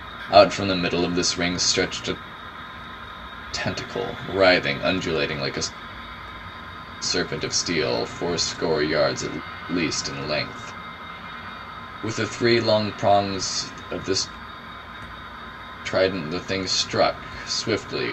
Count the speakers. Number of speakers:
1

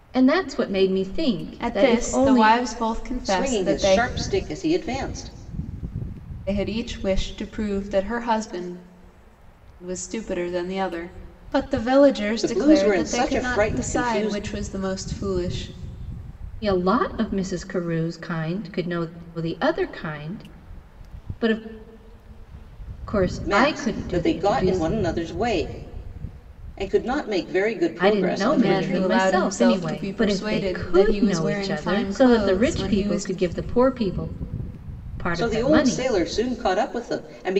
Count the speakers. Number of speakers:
3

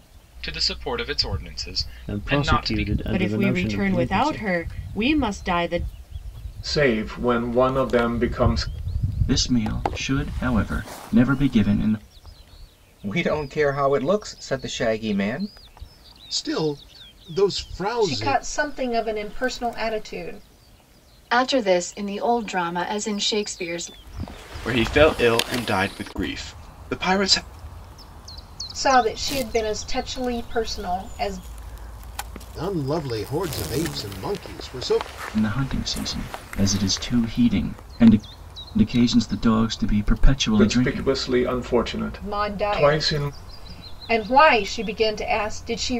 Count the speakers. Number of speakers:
10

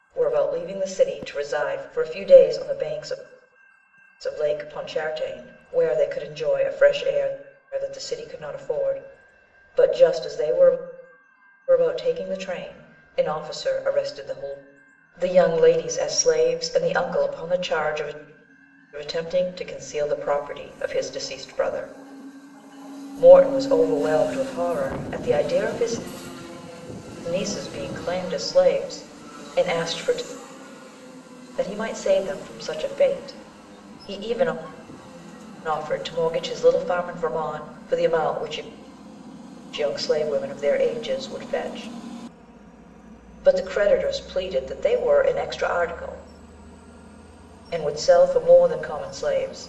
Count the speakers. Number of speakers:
1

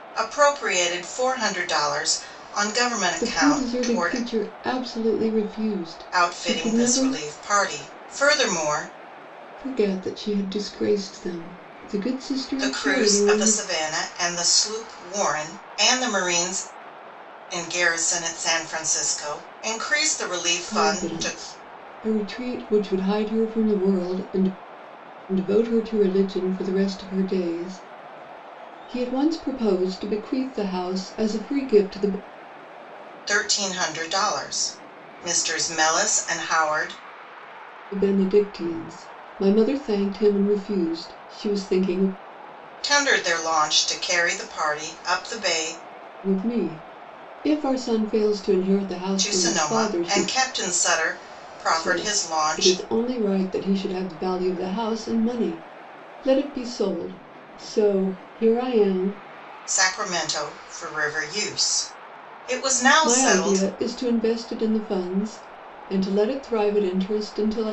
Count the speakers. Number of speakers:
2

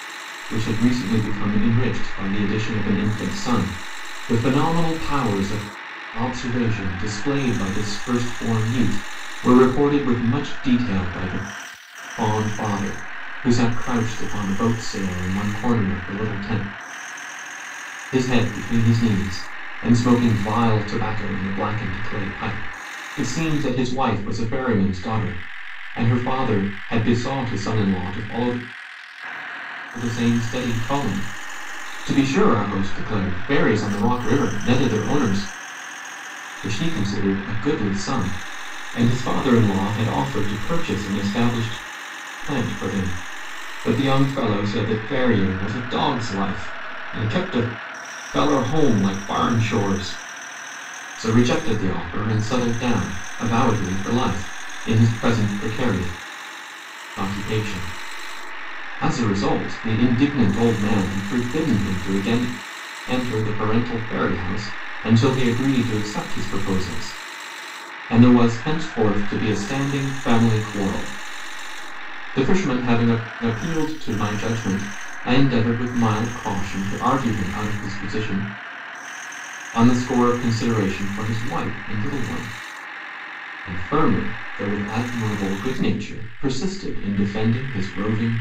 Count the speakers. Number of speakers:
1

